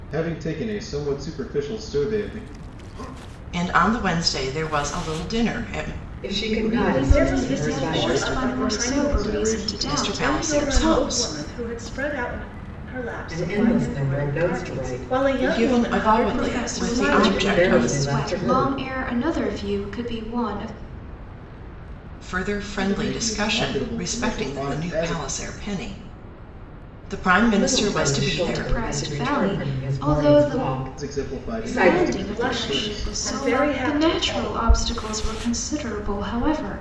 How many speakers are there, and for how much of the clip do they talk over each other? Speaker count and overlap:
5, about 53%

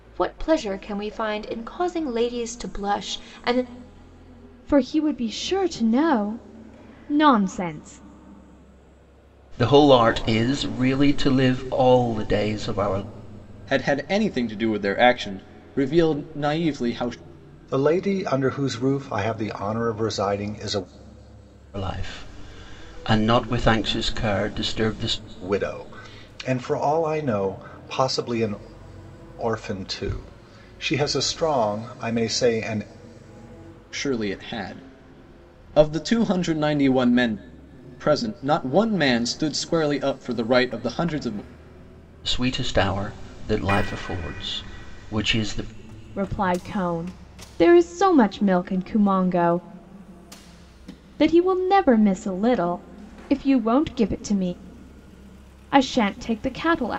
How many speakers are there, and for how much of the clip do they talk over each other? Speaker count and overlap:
5, no overlap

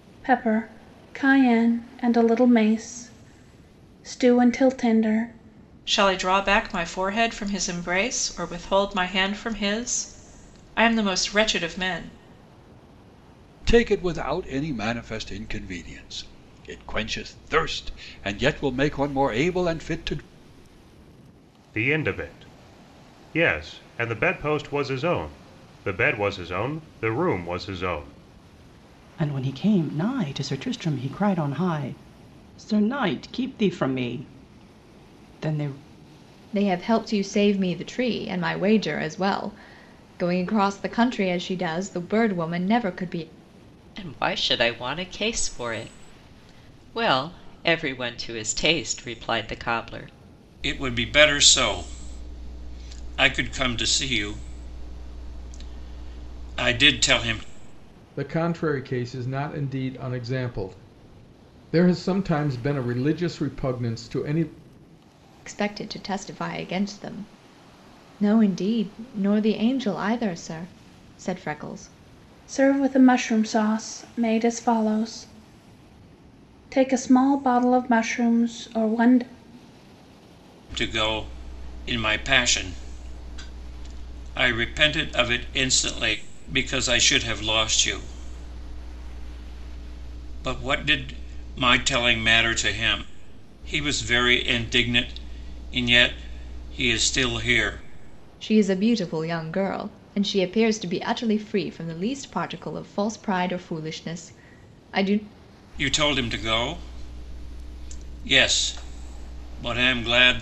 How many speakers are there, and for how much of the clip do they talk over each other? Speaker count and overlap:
9, no overlap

